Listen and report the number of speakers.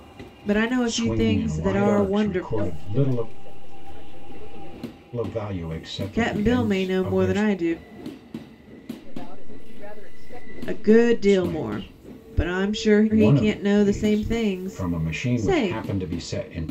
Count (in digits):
3